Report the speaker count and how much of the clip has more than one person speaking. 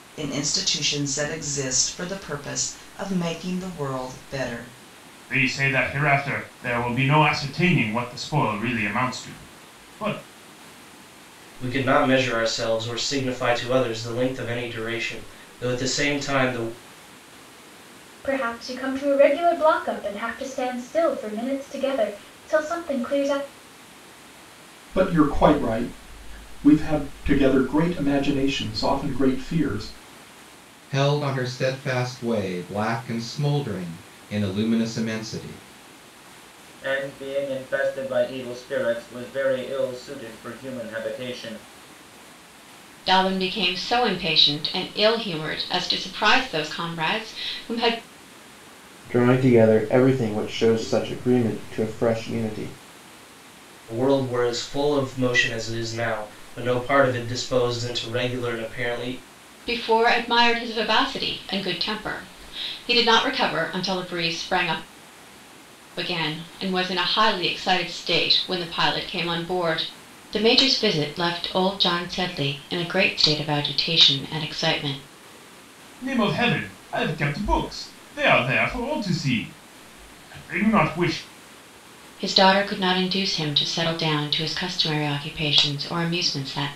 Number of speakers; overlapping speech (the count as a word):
nine, no overlap